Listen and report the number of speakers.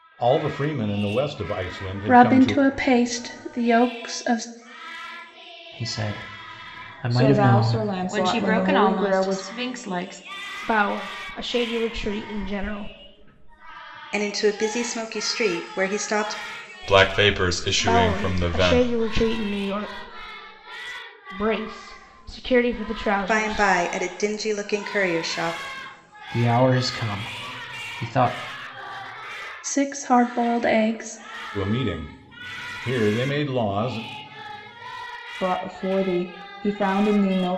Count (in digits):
8